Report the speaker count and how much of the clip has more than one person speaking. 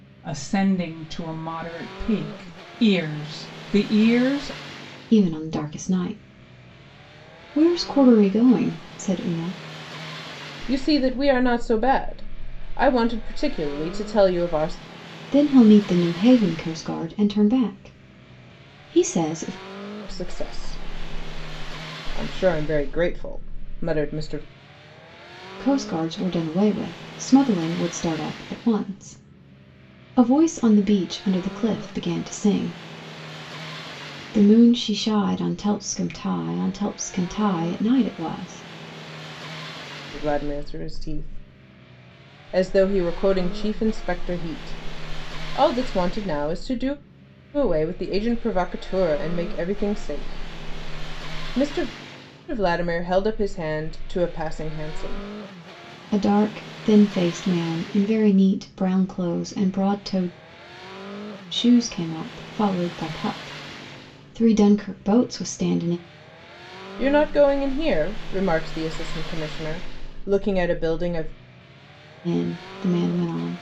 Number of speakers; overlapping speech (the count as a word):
three, no overlap